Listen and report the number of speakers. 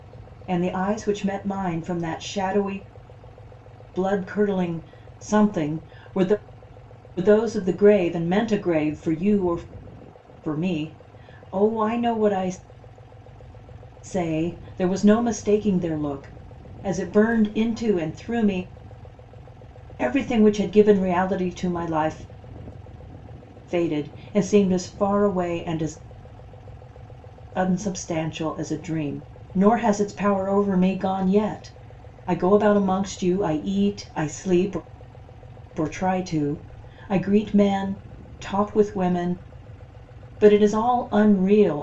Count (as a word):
one